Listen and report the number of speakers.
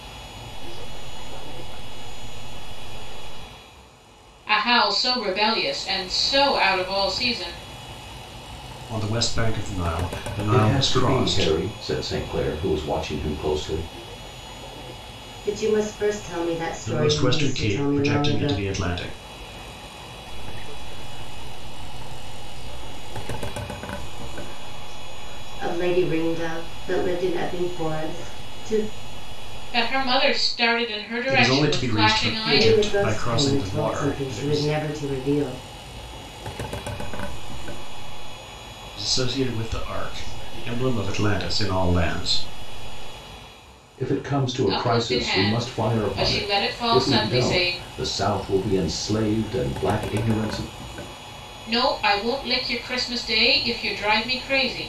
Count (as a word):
five